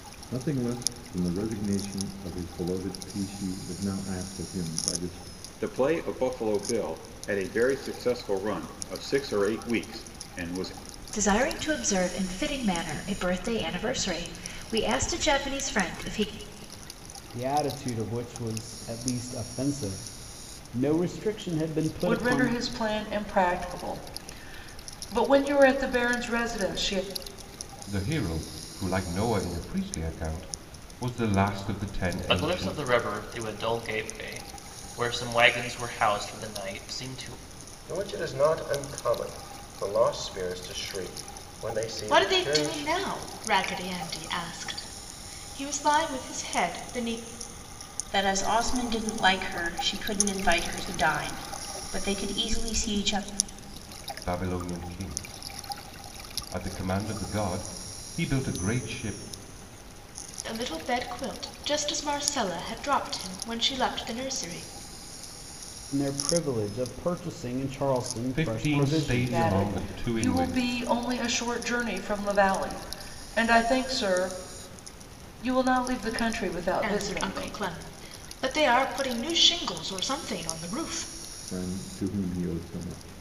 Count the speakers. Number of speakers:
ten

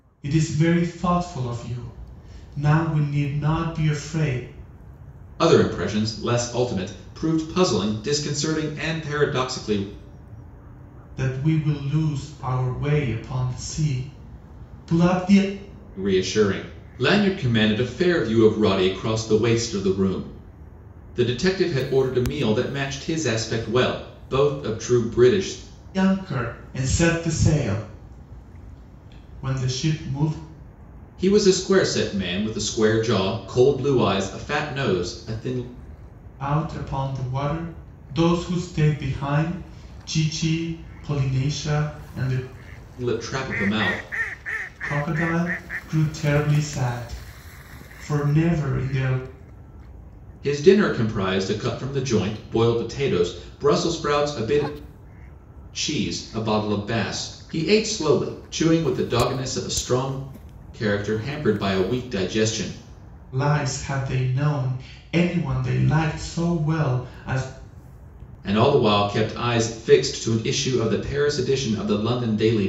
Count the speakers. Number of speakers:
two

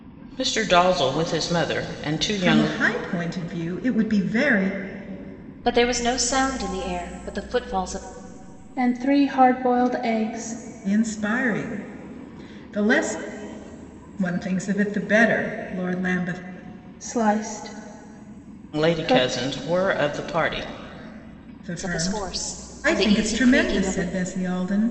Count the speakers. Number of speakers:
four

